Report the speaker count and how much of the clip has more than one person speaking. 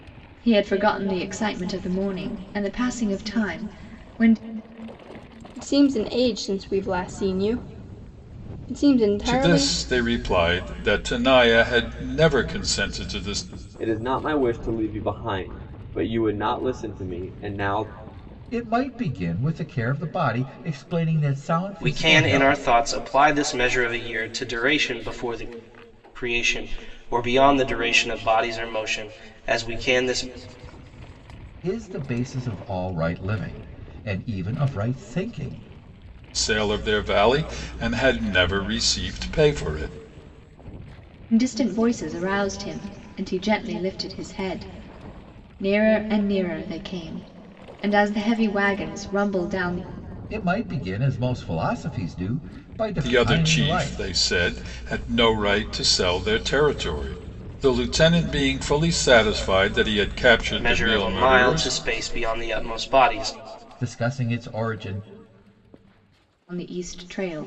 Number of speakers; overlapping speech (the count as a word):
six, about 6%